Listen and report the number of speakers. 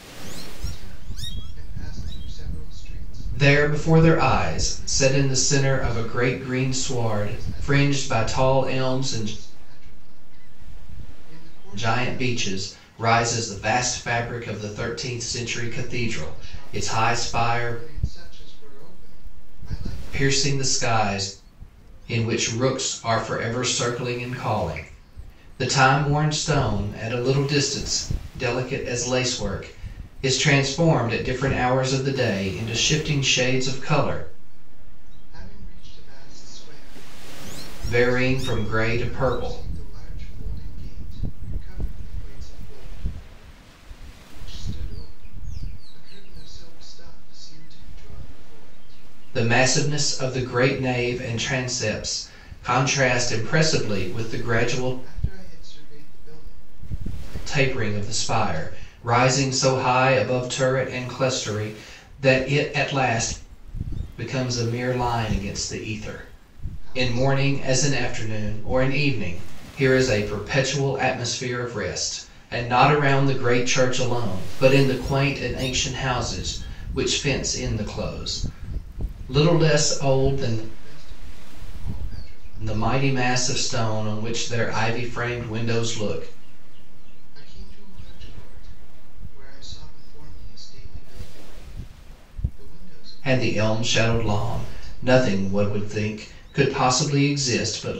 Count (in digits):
2